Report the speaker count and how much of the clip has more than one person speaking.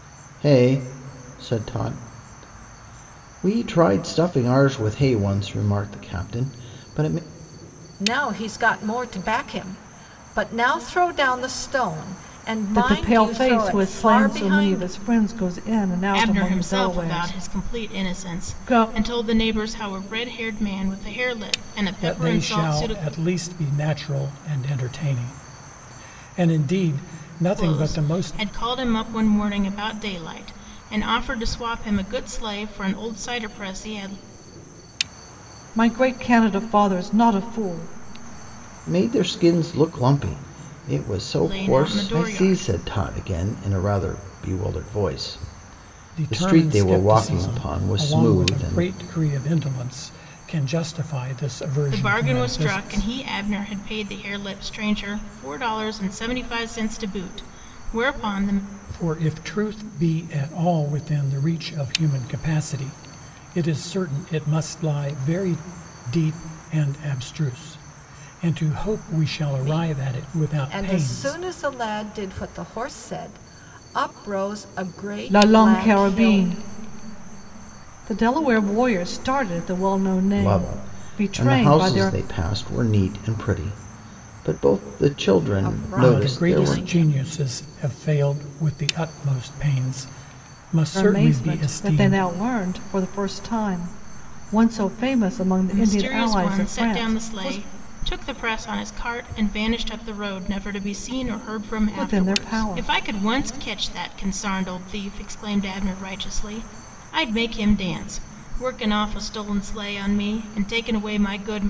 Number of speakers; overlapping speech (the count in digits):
5, about 21%